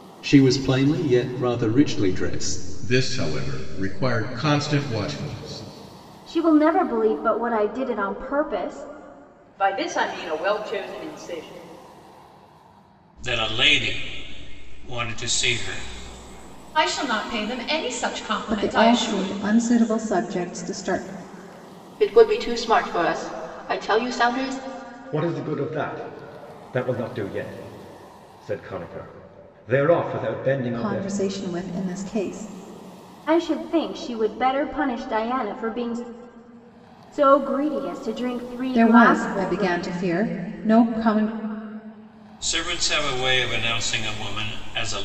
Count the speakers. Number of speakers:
10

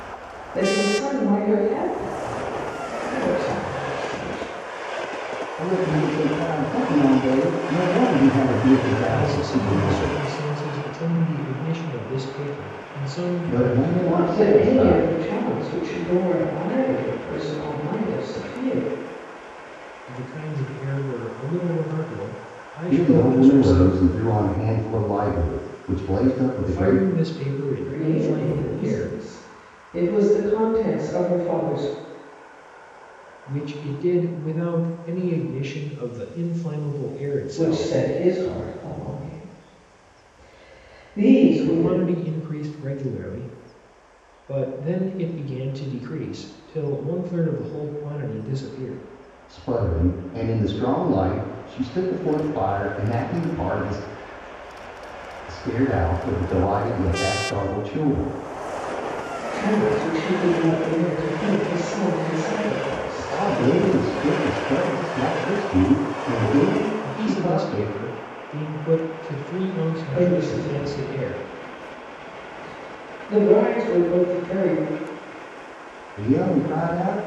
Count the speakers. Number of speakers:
3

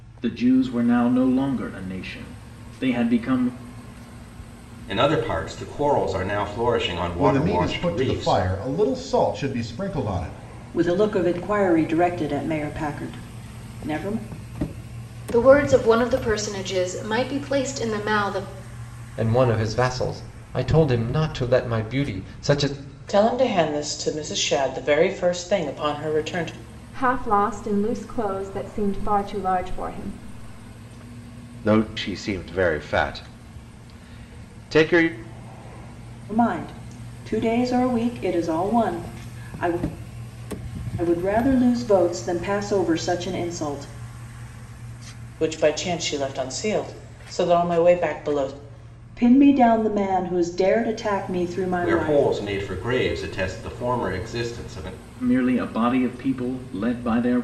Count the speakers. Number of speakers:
9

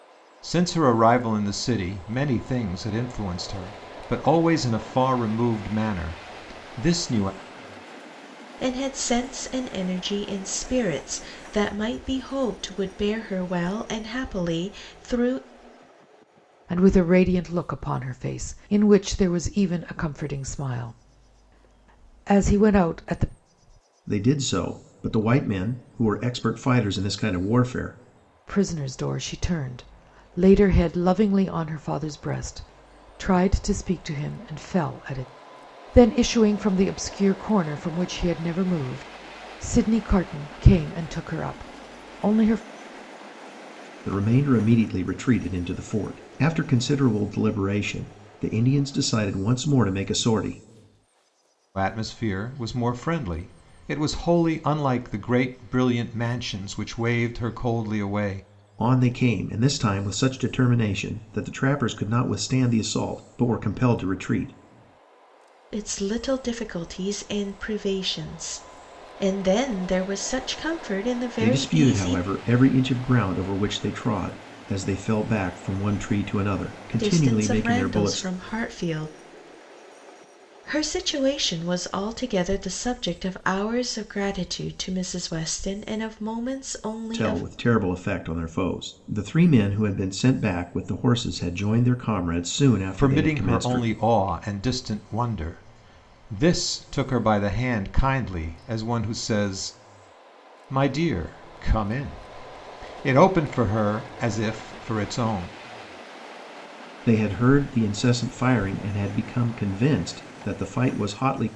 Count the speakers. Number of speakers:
4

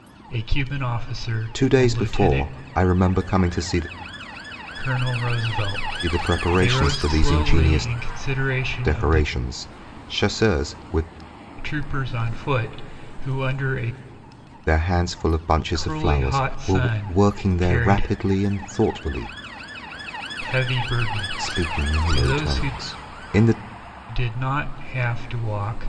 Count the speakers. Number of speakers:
2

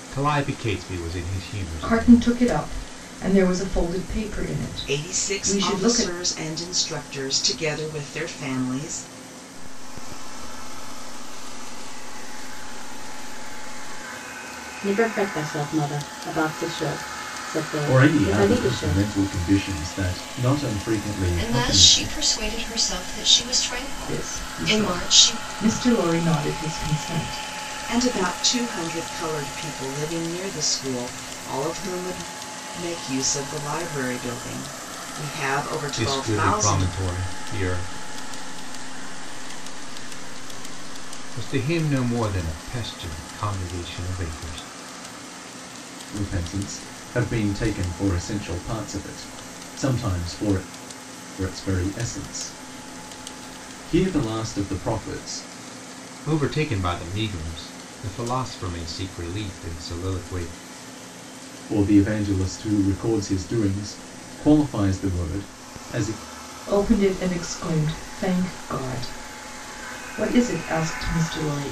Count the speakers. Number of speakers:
7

